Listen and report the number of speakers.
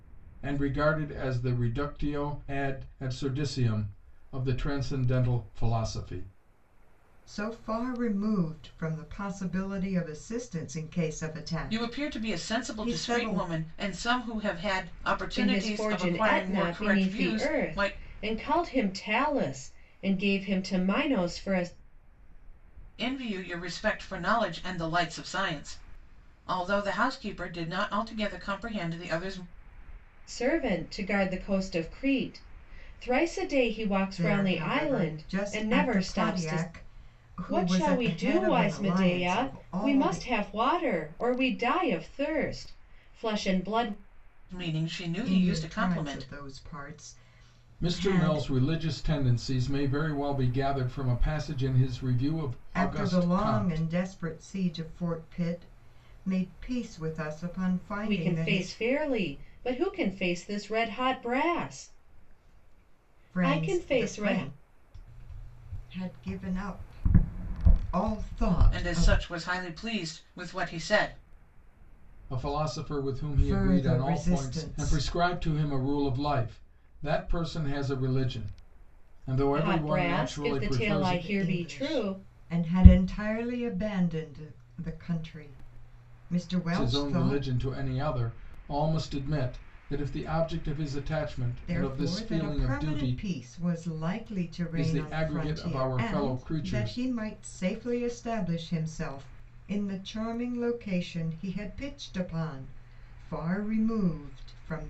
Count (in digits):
4